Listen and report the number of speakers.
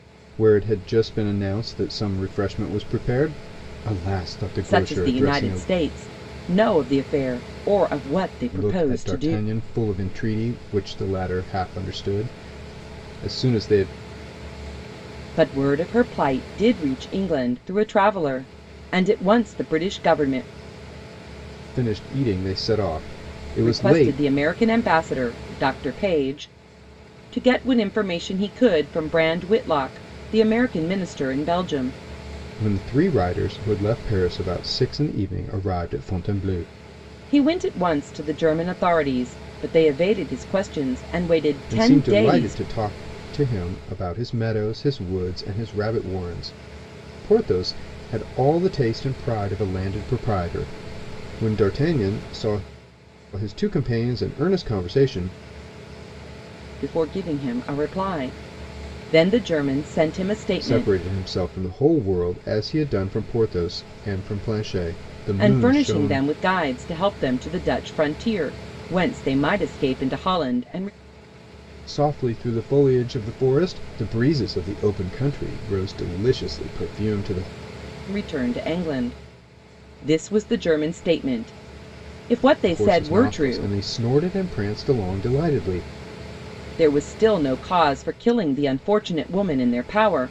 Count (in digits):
2